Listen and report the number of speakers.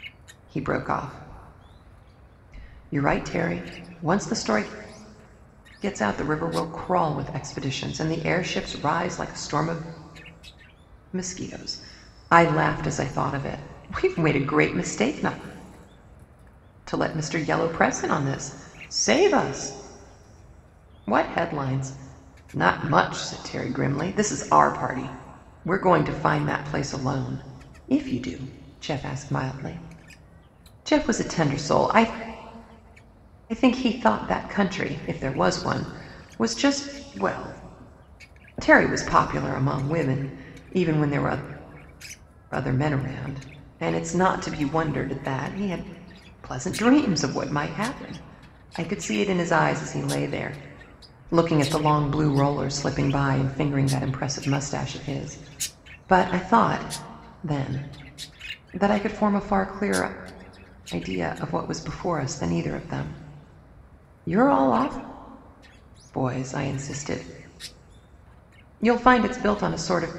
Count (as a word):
one